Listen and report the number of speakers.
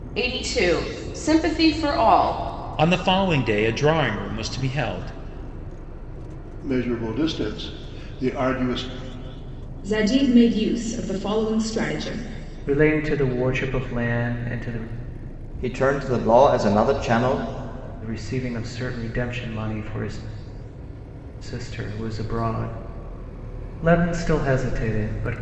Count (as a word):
six